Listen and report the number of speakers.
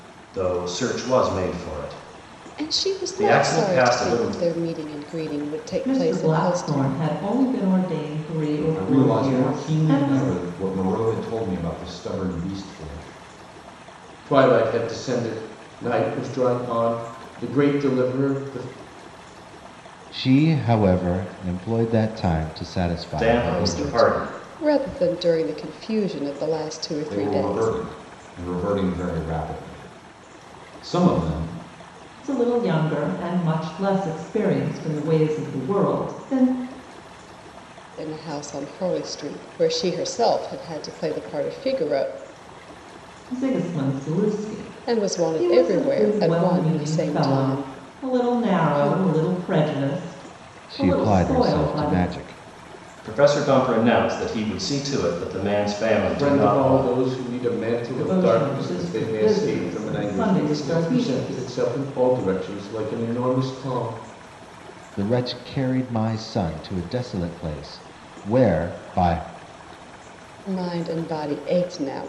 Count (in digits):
6